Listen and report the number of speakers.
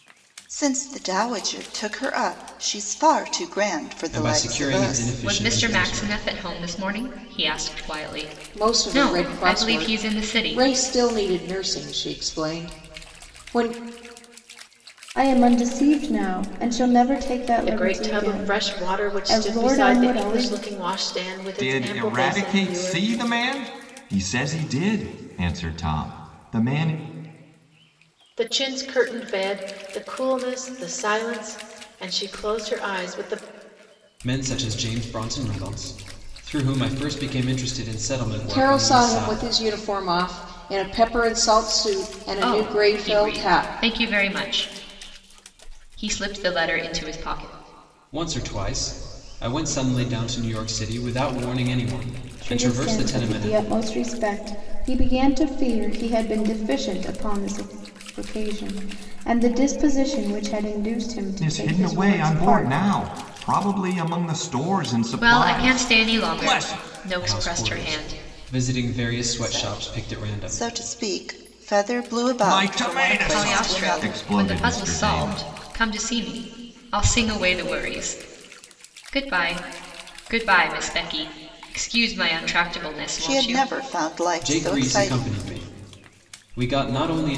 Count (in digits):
7